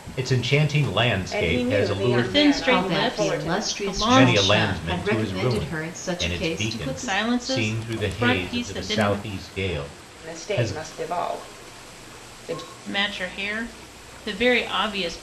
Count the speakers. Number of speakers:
4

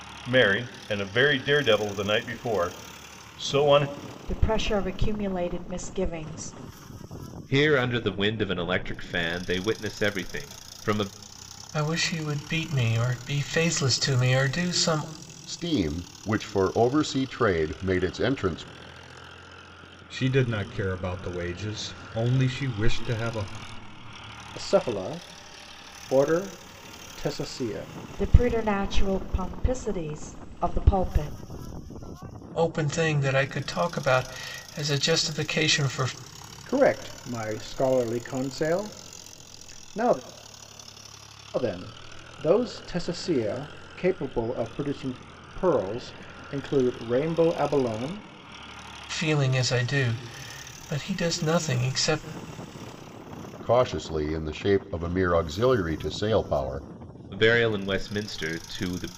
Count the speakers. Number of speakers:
7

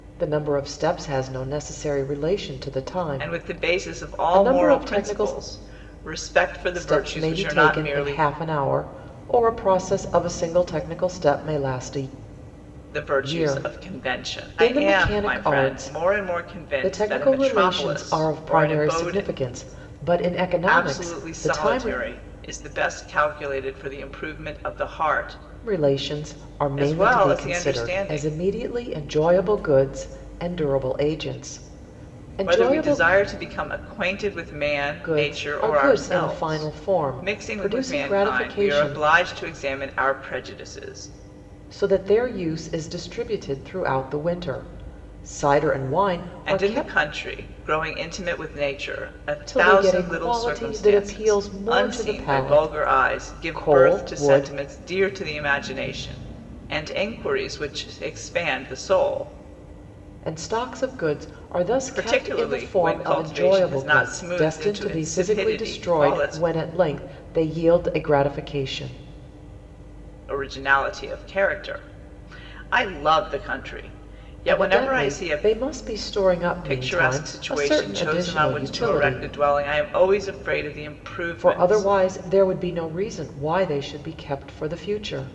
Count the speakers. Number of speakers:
2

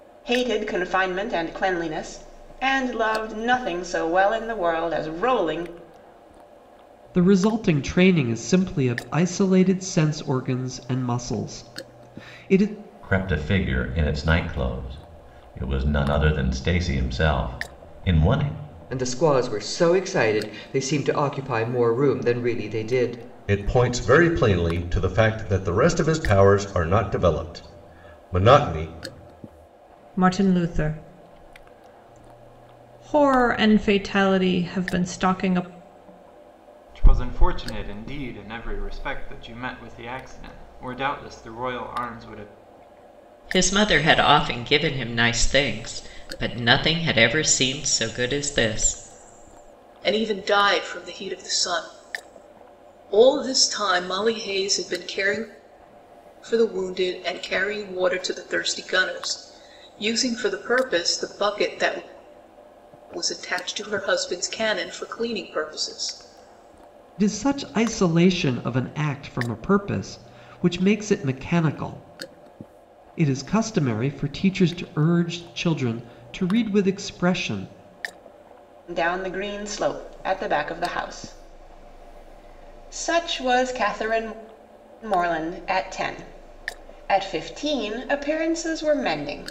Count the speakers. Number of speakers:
9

